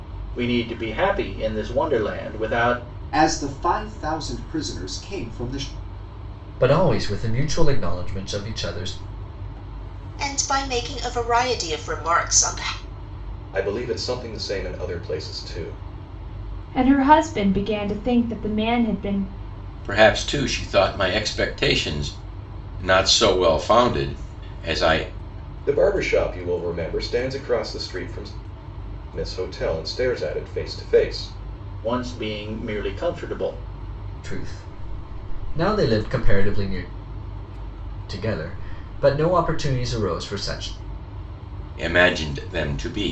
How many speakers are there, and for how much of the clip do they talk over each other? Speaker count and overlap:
7, no overlap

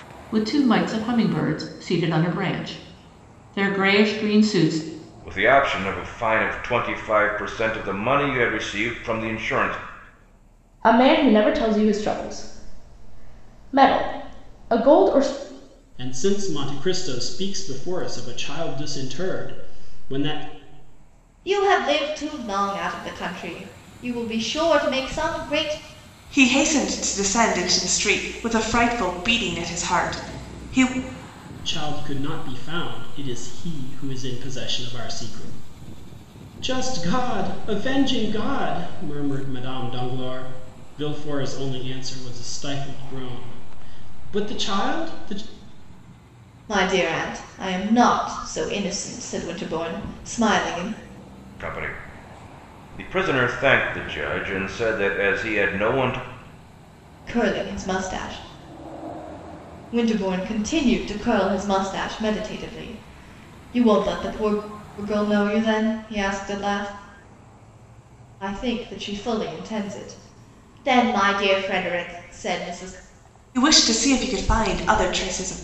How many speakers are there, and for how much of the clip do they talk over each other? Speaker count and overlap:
6, no overlap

